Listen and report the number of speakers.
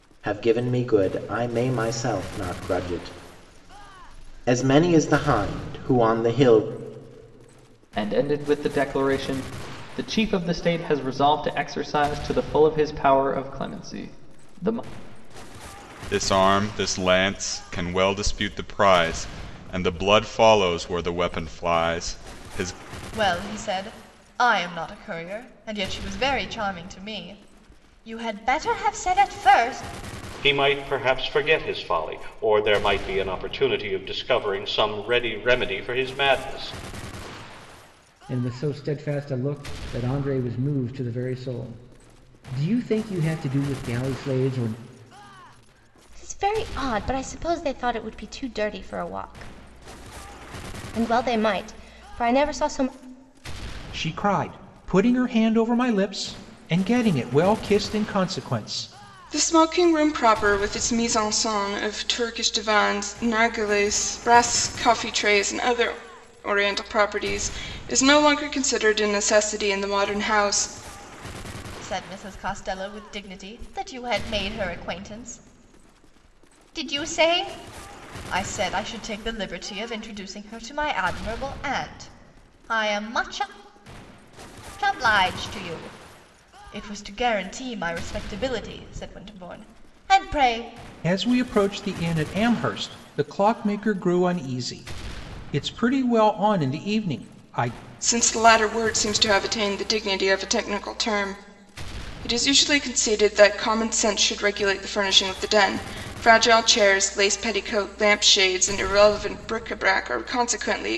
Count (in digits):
9